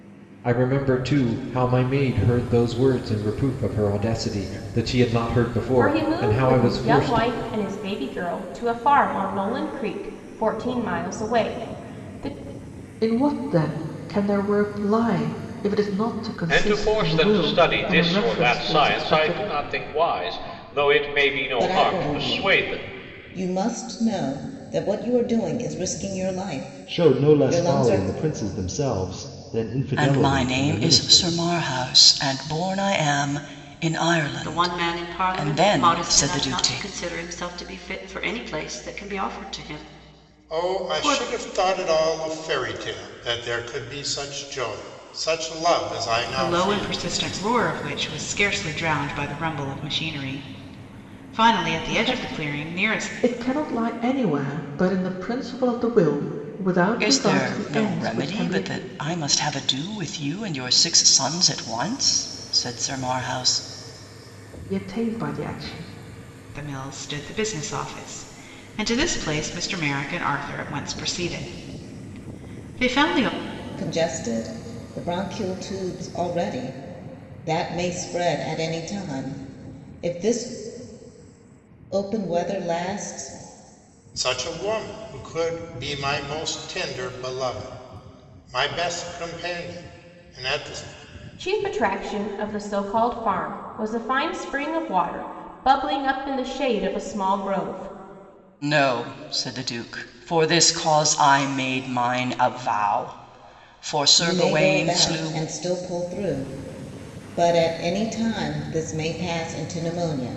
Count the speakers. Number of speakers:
10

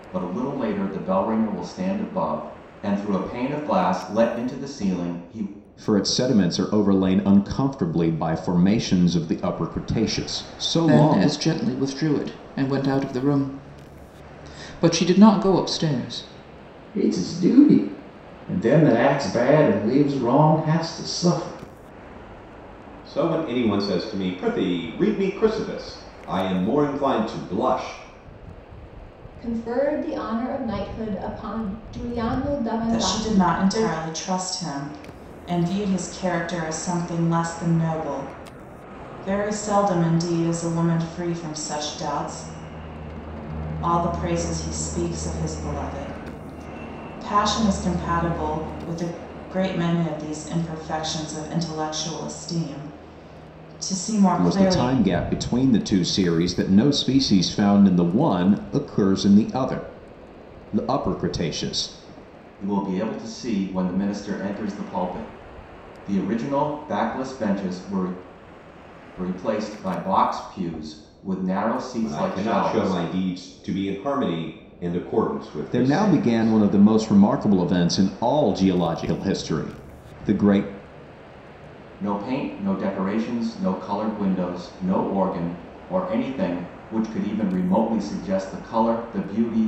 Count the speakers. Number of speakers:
7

